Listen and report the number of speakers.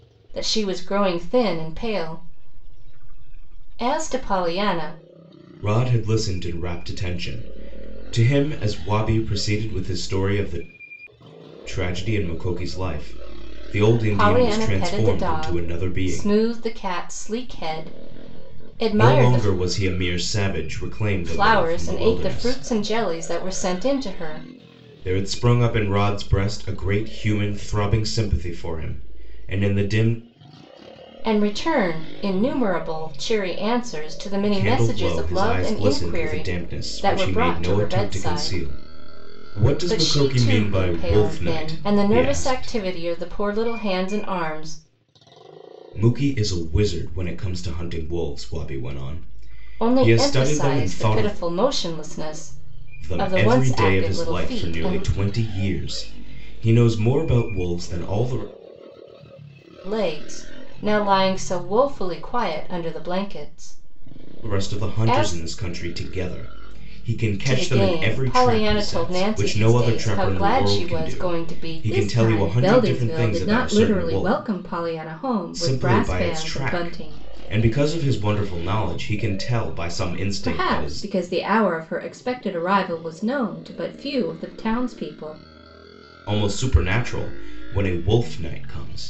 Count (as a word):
two